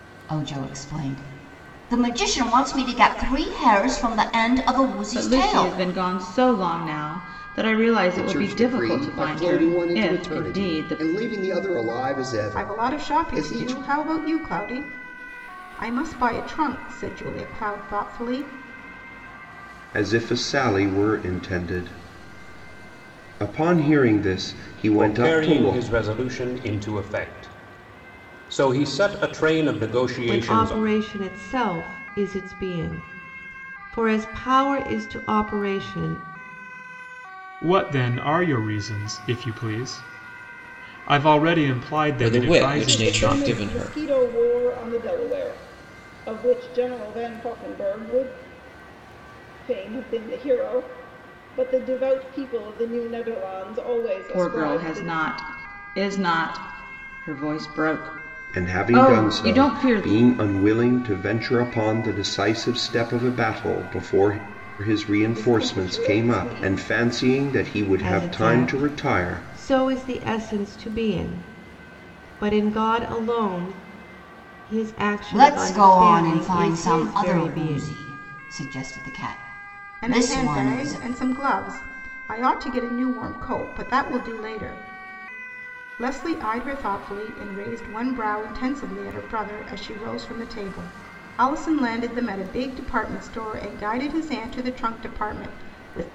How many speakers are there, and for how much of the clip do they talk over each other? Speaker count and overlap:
ten, about 19%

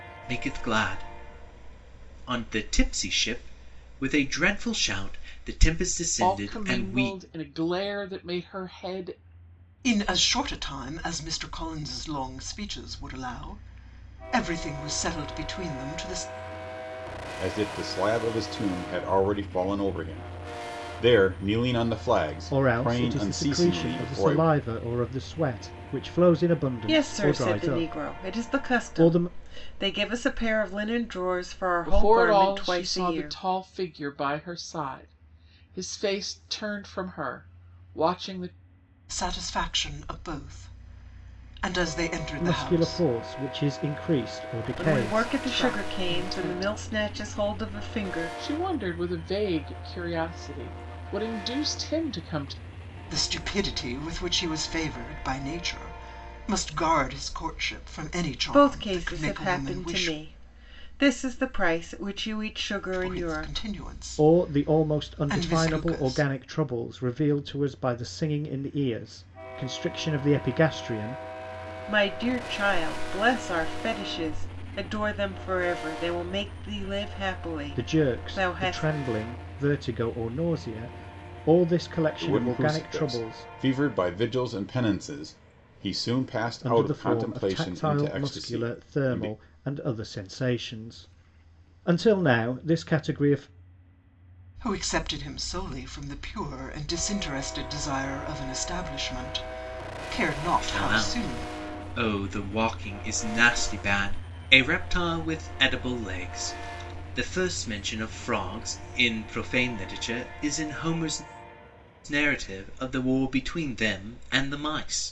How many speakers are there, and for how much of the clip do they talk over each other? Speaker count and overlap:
six, about 19%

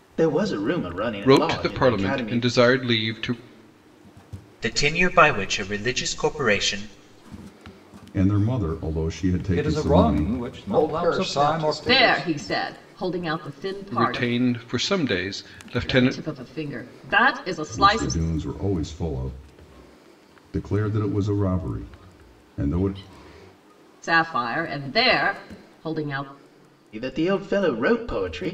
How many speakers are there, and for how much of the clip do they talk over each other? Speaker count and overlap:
seven, about 17%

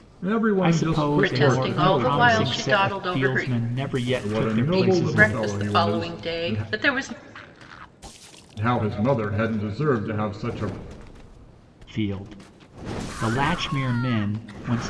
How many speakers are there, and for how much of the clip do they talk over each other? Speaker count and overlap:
three, about 36%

